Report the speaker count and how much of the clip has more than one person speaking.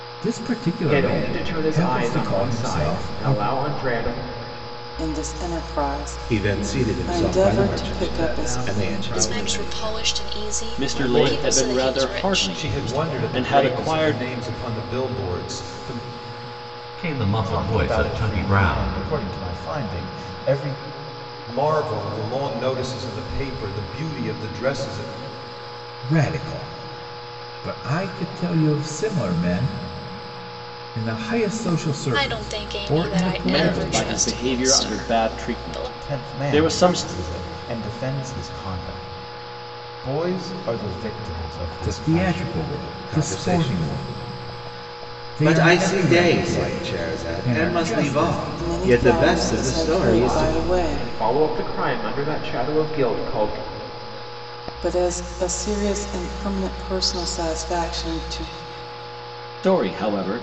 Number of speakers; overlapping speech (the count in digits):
10, about 42%